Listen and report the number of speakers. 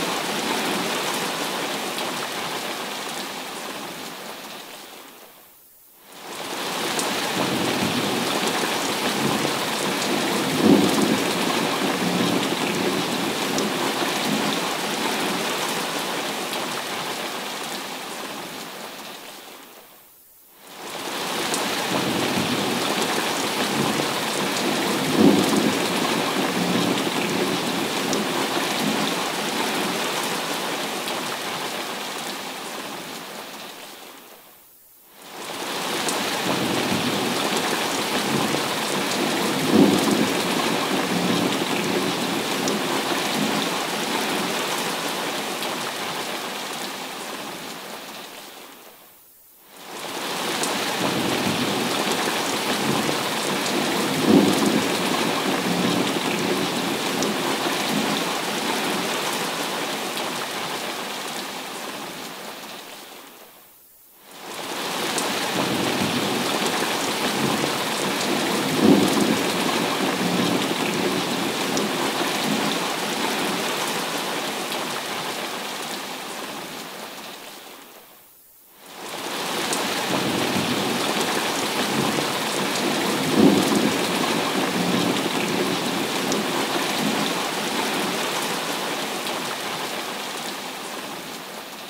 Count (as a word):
zero